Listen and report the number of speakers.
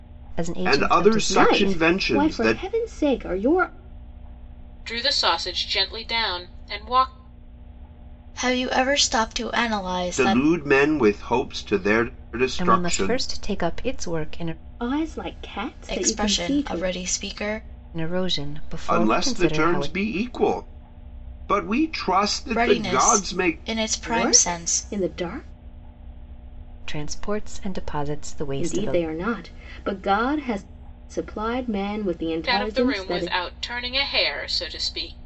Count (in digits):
5